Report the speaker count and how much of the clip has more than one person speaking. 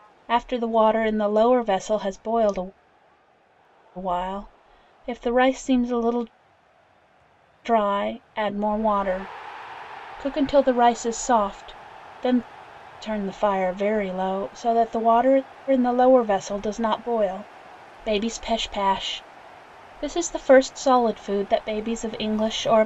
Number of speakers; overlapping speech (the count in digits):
1, no overlap